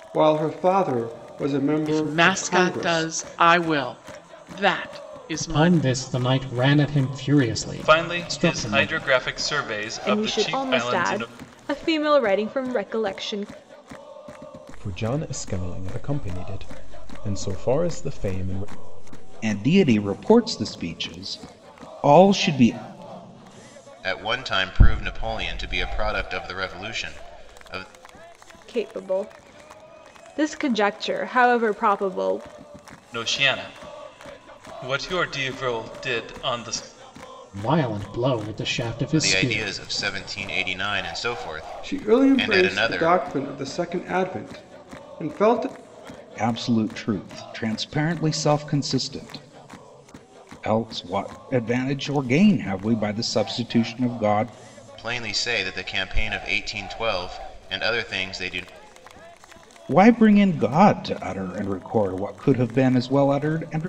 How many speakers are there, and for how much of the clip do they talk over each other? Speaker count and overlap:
8, about 9%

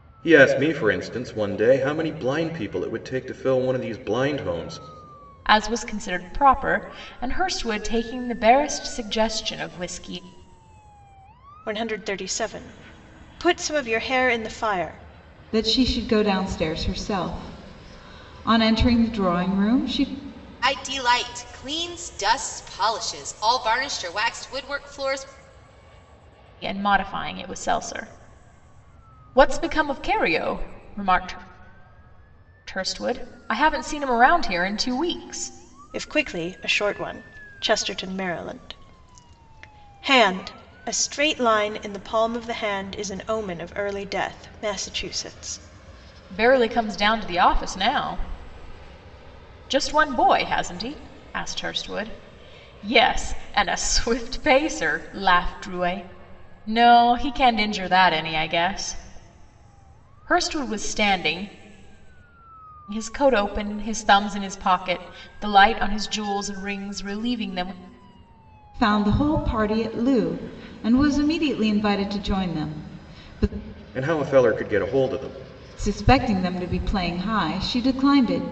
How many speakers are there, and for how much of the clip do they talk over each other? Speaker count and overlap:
5, no overlap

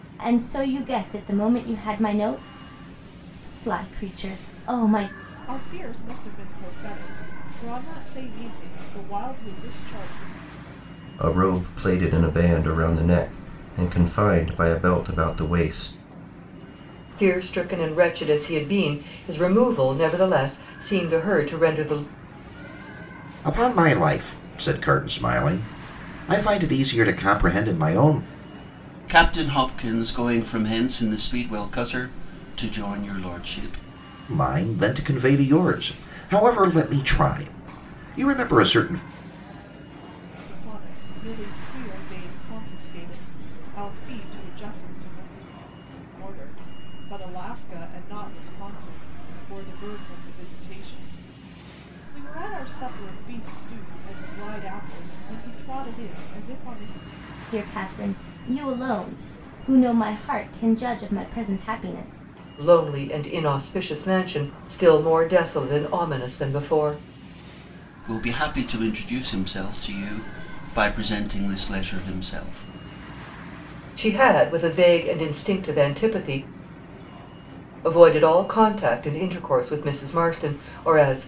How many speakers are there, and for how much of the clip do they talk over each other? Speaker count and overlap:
6, no overlap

